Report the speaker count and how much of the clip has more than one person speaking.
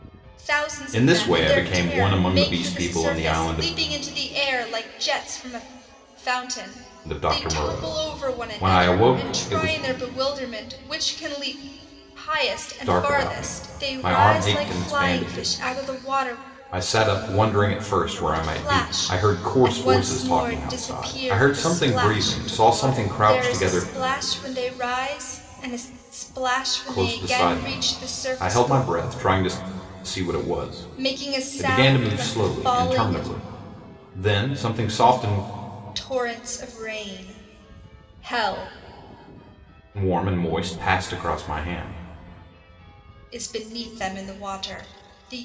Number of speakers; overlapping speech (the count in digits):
2, about 40%